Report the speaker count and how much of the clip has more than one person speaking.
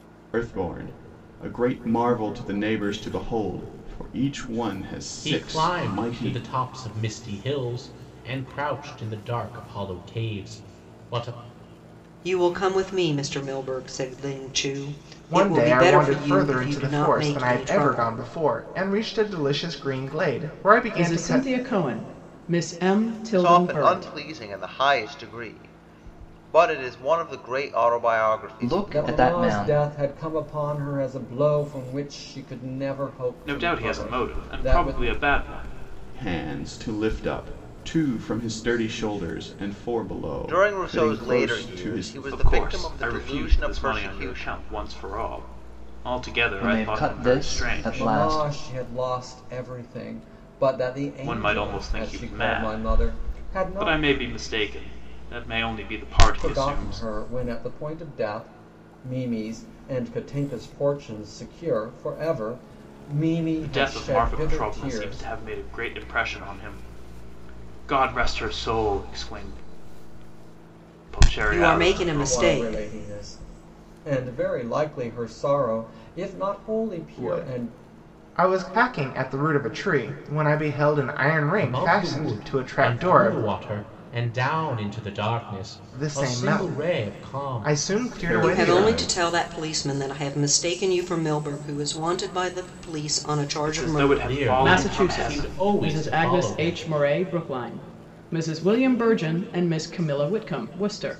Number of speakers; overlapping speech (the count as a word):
nine, about 30%